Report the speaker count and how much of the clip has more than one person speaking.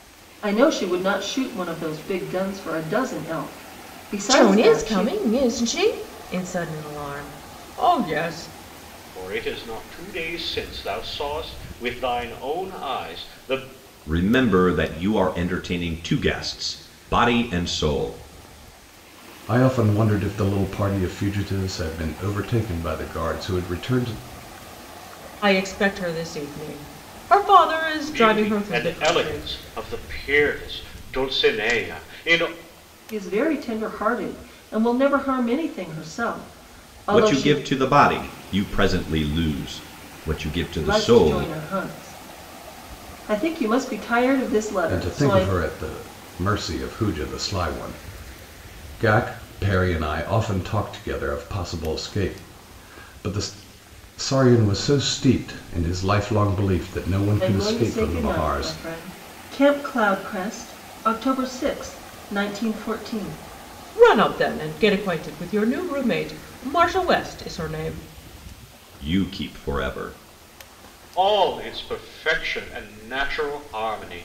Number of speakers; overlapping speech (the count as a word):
five, about 7%